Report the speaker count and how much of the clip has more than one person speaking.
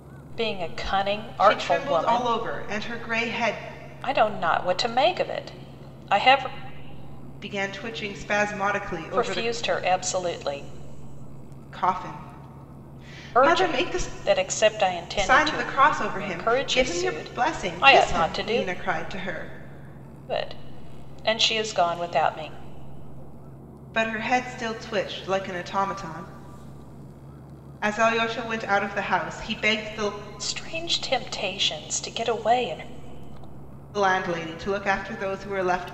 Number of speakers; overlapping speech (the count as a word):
two, about 14%